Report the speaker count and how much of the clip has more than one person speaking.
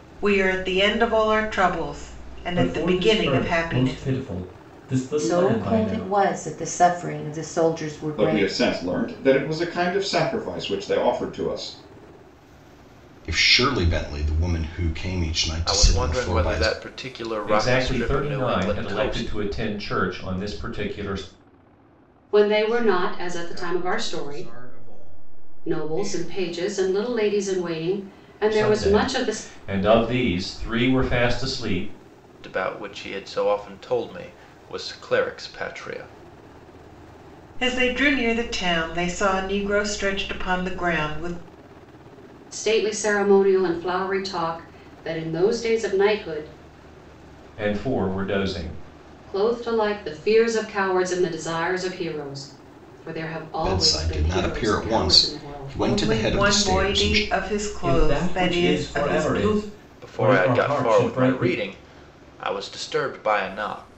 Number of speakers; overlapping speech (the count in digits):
9, about 26%